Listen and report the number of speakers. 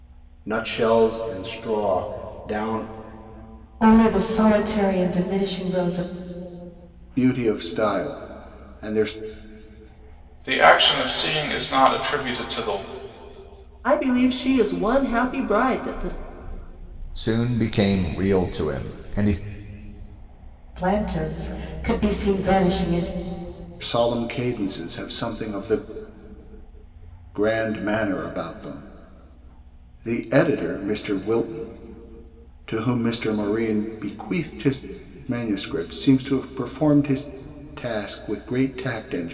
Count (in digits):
6